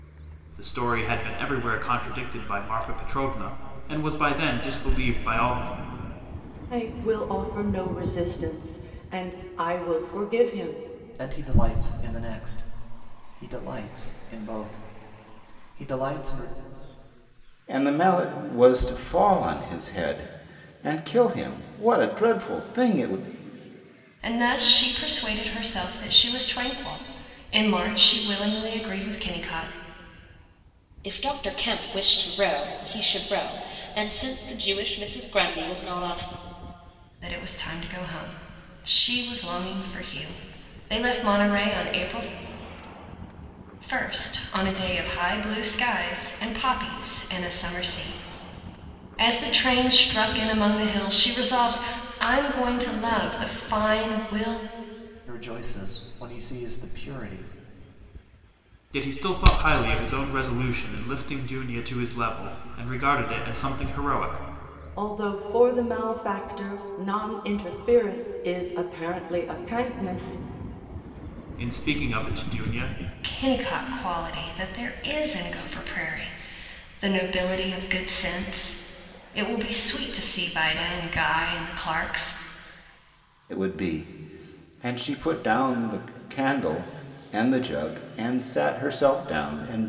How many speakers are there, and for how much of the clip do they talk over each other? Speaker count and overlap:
6, no overlap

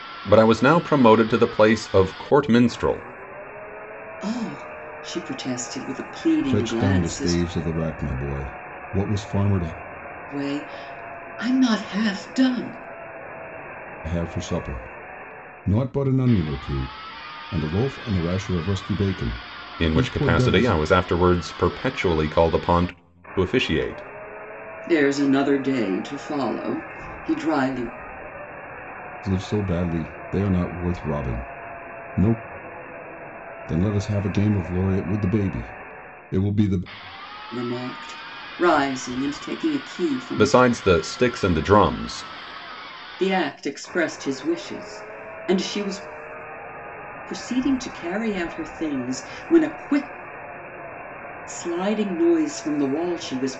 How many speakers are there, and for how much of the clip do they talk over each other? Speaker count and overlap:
3, about 4%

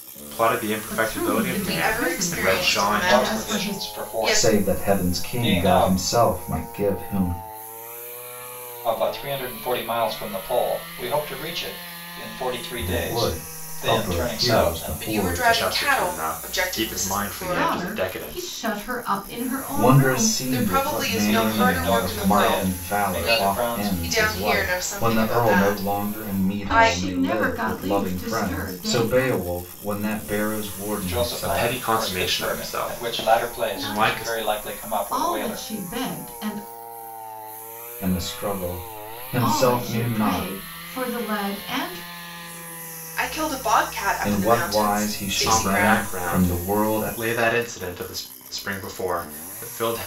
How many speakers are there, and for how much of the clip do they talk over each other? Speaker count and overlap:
5, about 58%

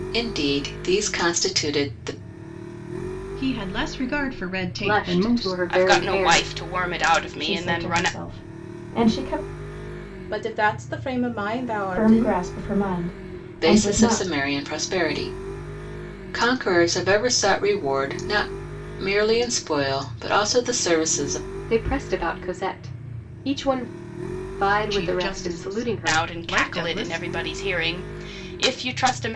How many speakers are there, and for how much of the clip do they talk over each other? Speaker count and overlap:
6, about 21%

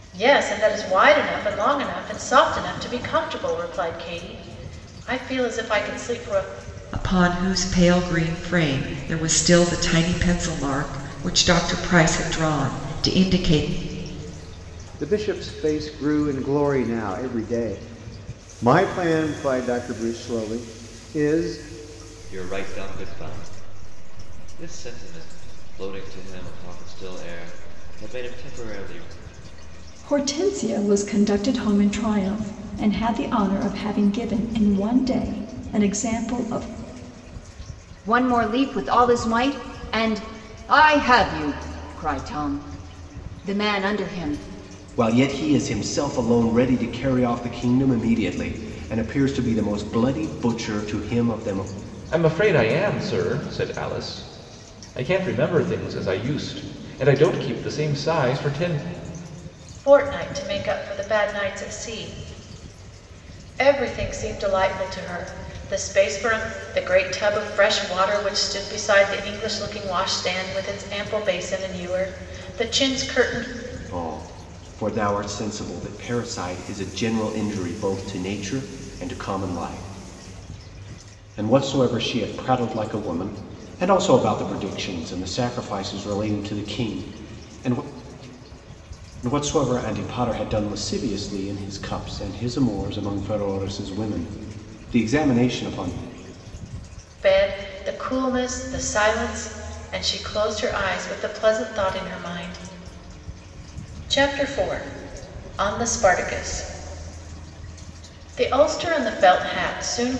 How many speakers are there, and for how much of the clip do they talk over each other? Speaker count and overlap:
8, no overlap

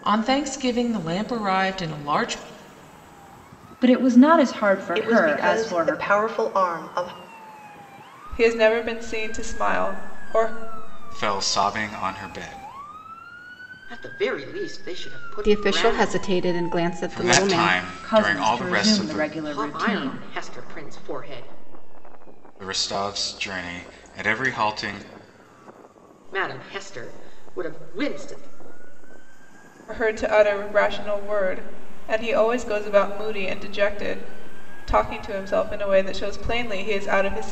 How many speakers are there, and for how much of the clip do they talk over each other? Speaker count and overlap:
7, about 13%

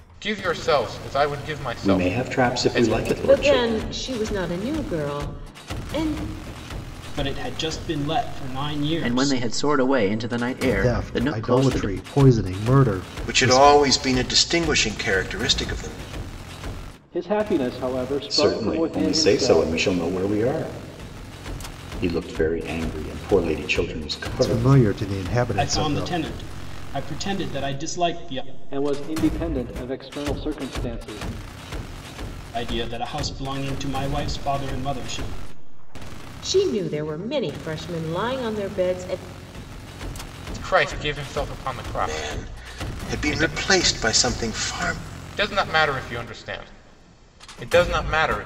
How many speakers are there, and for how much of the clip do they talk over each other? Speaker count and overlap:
8, about 16%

